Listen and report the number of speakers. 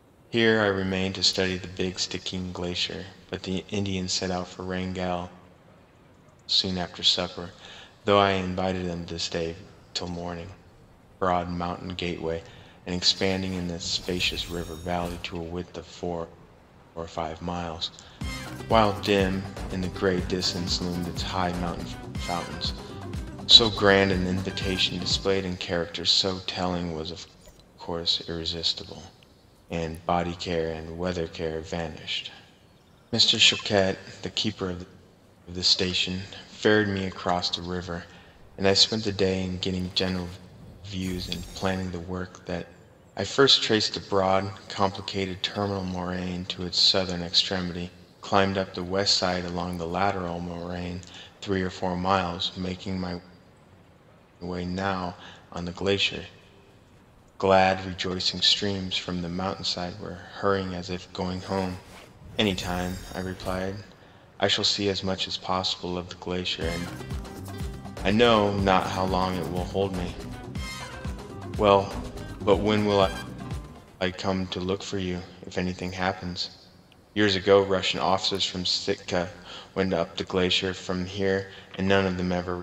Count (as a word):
one